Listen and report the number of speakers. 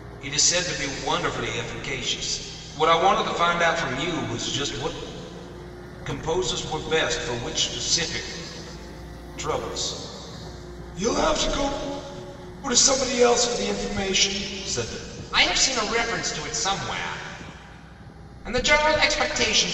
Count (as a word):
one